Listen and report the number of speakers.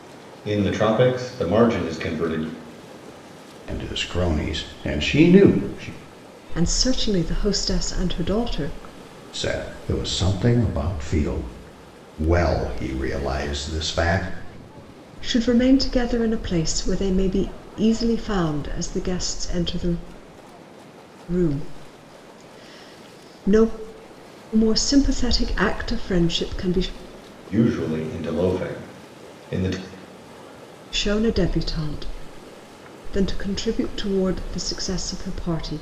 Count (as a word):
three